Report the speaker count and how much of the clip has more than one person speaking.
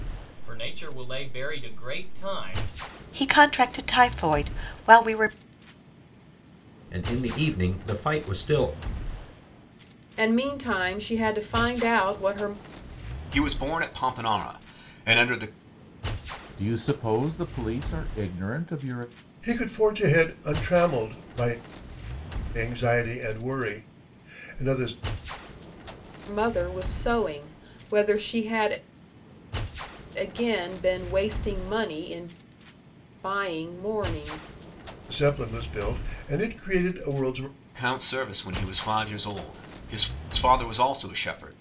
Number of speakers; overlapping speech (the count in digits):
7, no overlap